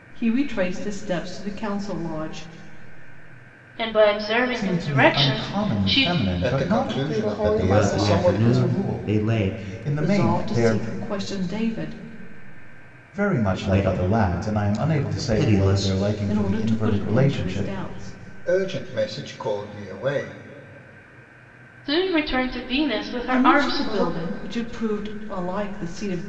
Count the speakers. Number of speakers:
6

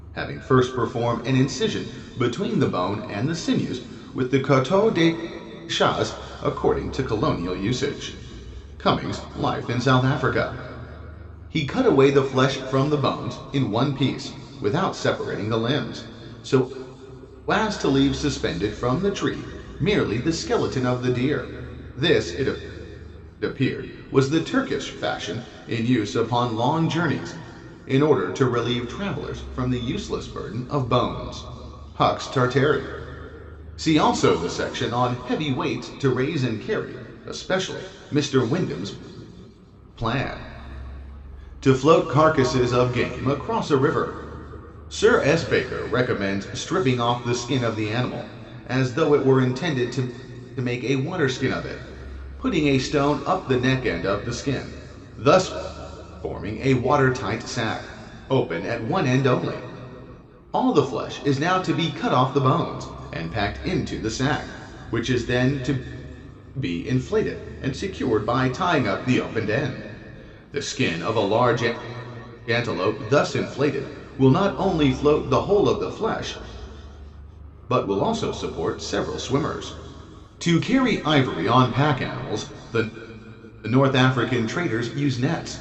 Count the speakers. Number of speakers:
1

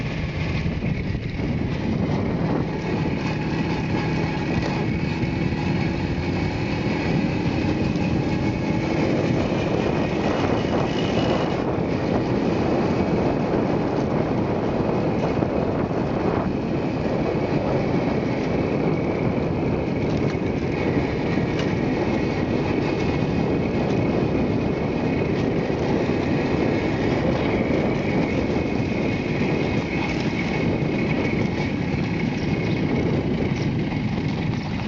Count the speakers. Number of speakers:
0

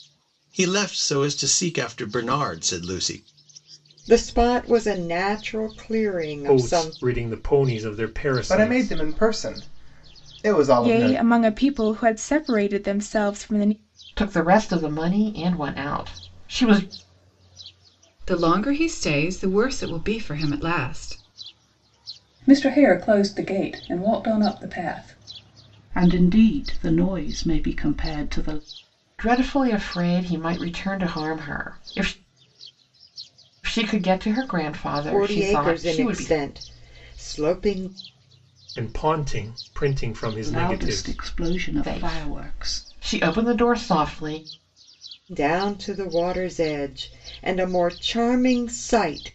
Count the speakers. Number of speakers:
9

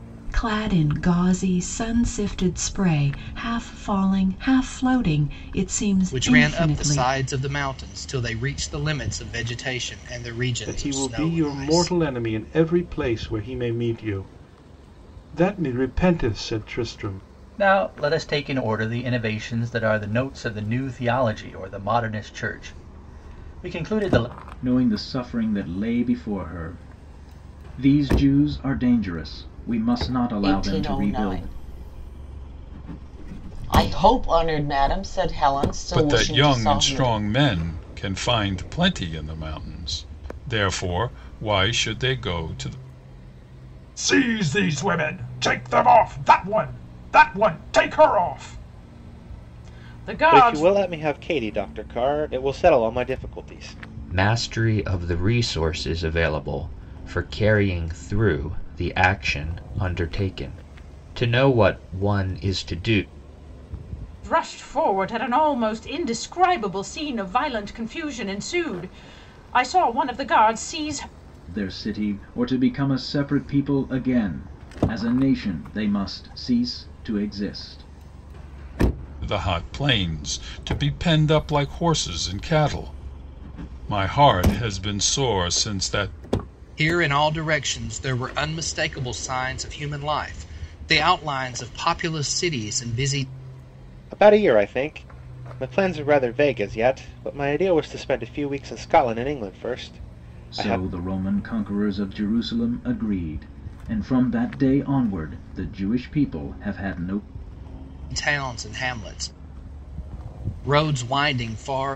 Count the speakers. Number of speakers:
10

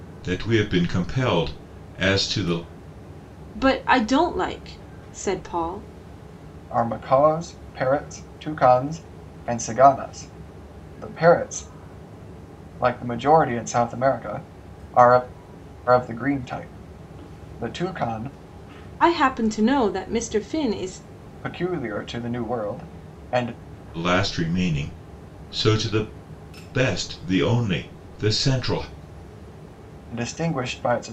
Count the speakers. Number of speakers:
3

